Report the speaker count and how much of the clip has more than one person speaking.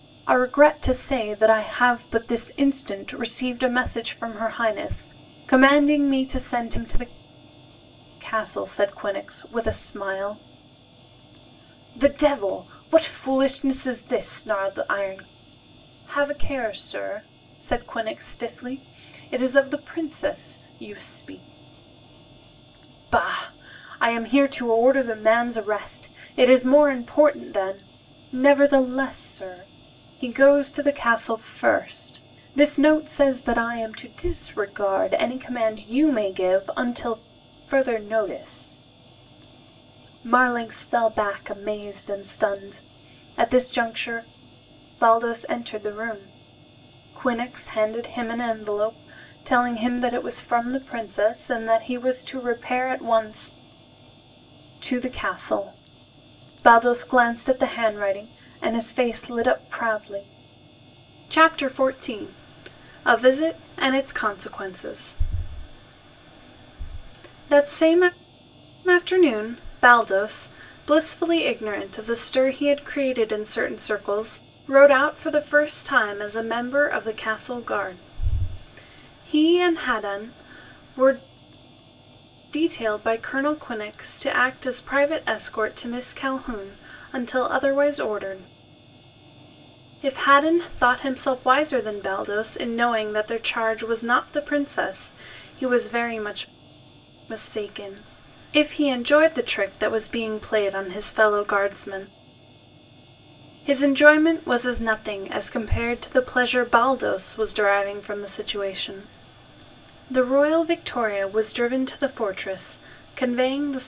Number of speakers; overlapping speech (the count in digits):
1, no overlap